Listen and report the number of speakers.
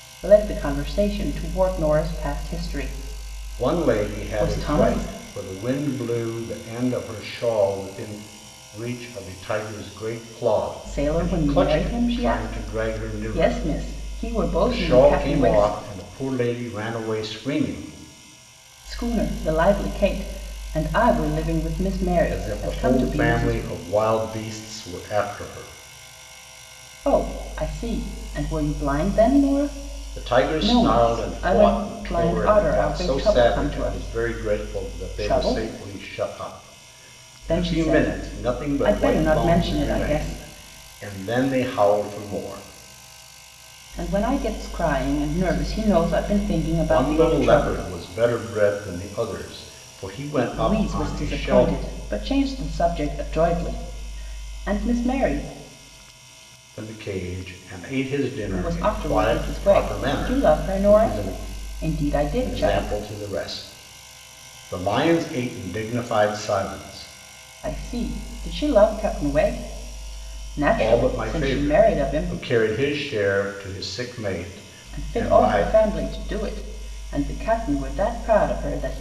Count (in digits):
2